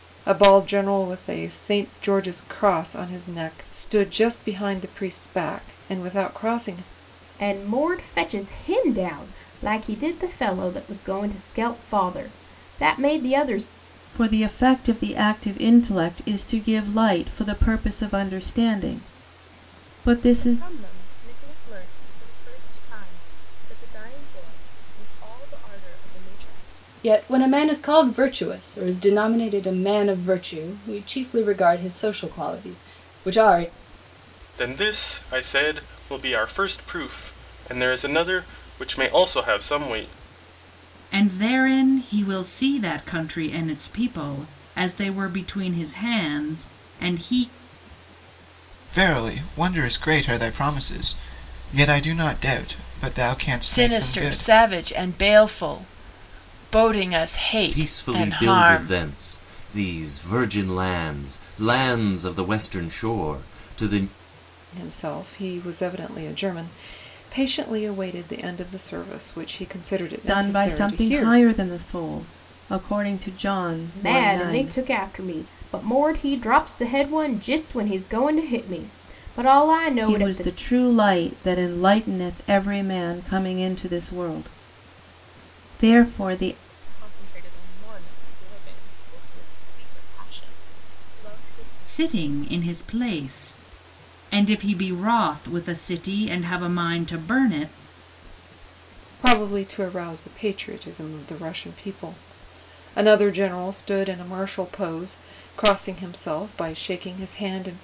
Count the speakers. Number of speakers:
10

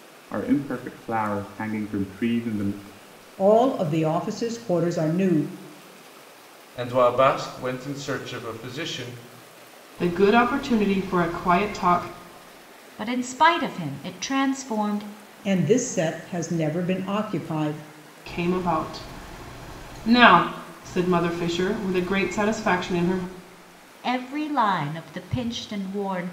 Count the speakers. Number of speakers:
5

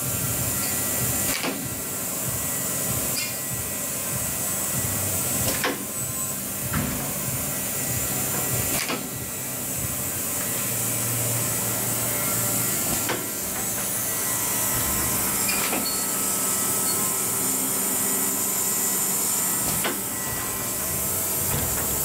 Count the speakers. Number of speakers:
0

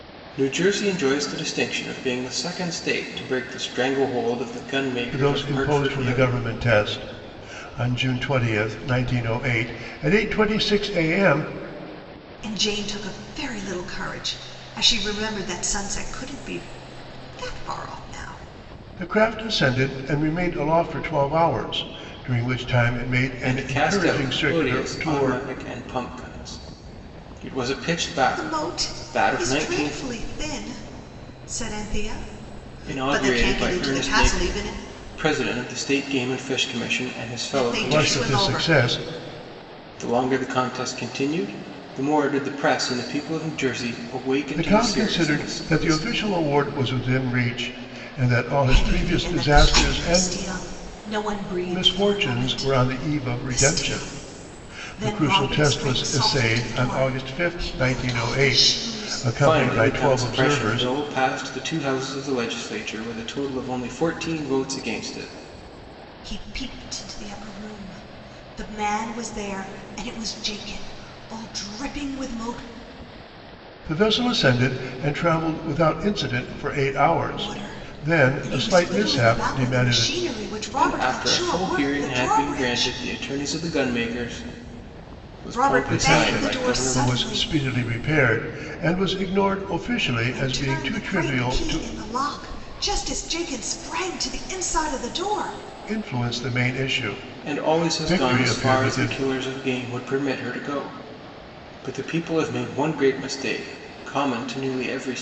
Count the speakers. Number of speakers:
3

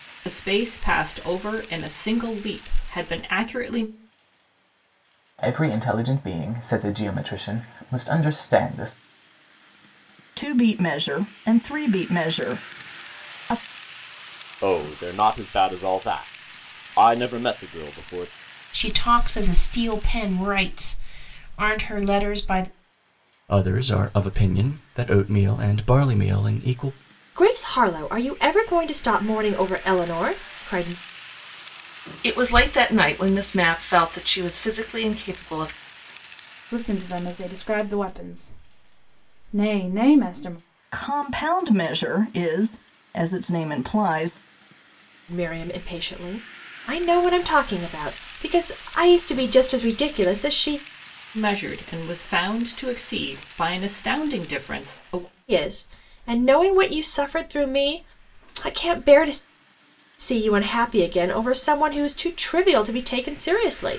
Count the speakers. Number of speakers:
9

